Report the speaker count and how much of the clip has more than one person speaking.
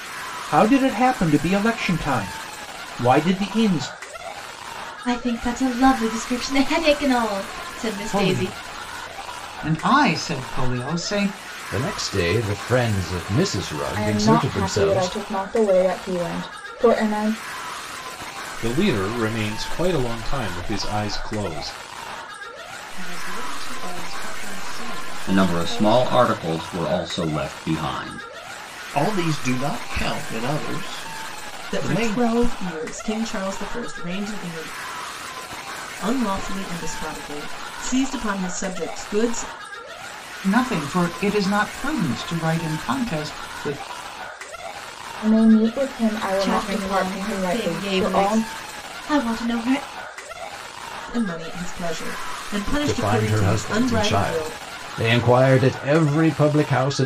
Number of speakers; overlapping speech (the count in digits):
10, about 13%